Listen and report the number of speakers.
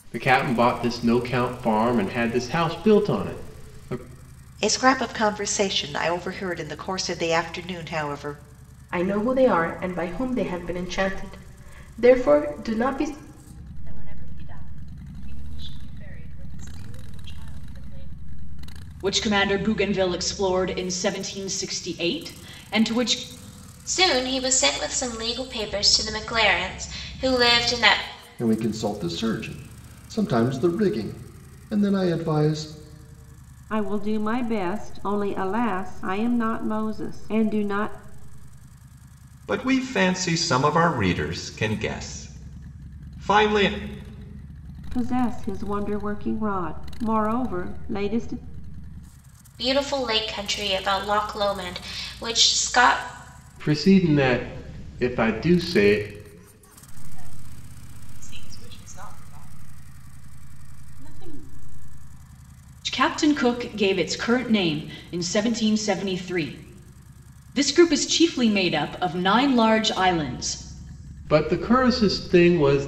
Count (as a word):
nine